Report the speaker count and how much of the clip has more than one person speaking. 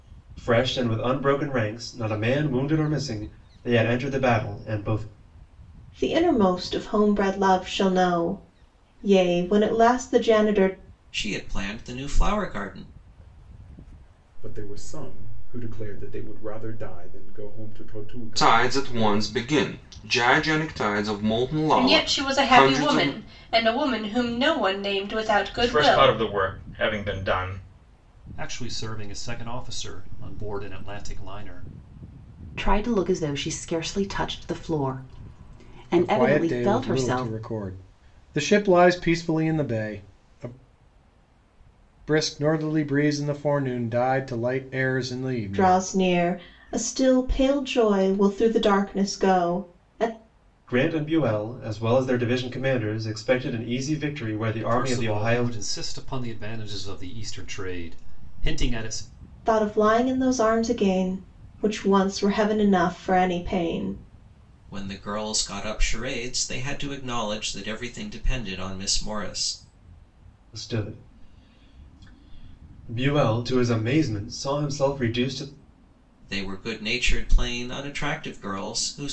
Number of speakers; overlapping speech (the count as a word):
ten, about 7%